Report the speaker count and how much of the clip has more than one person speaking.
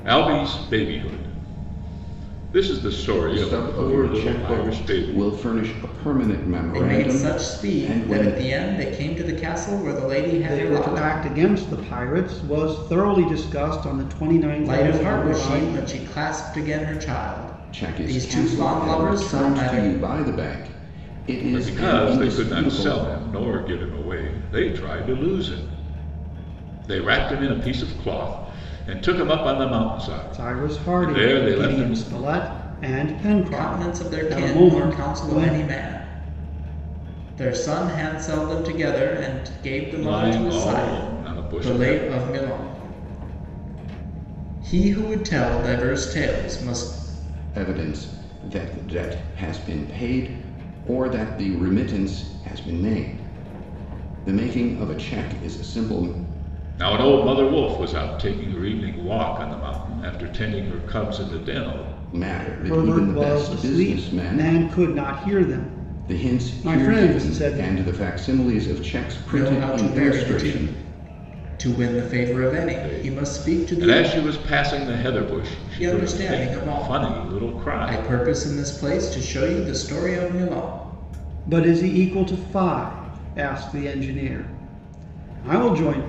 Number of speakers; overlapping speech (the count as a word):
four, about 27%